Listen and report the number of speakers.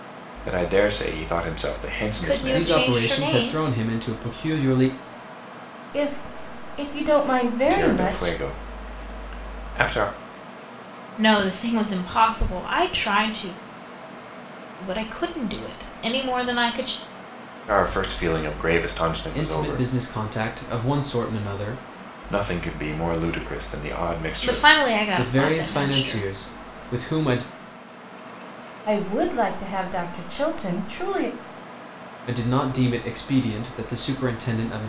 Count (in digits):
4